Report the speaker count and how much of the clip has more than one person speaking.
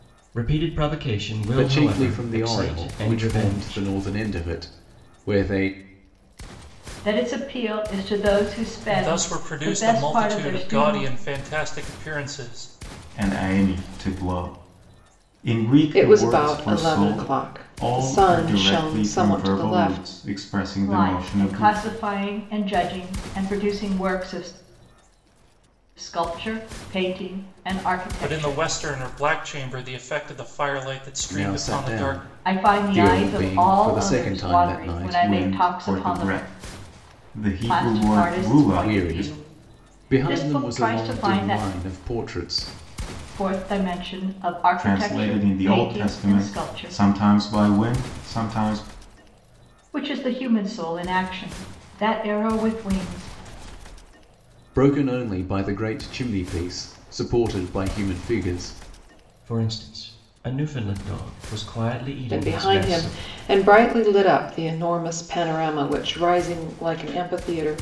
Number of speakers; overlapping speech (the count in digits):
6, about 33%